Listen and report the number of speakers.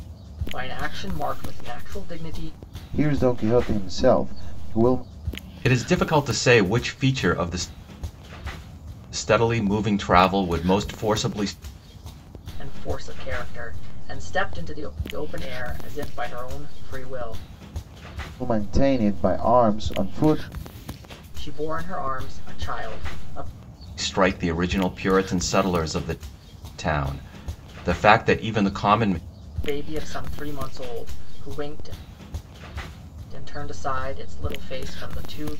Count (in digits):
3